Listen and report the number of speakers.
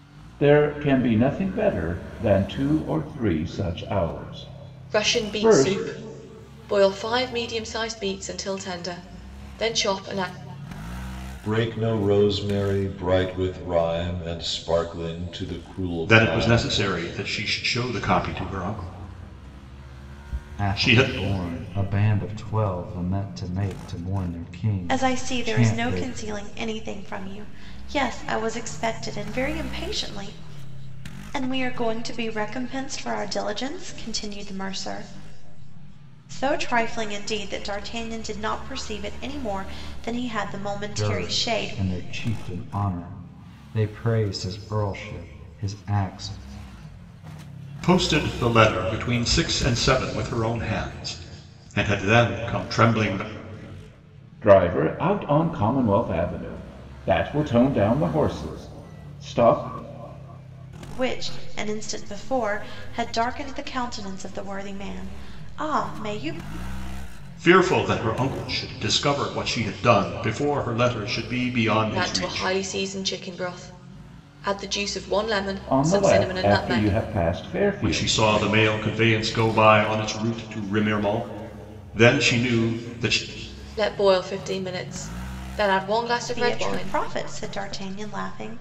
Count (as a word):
six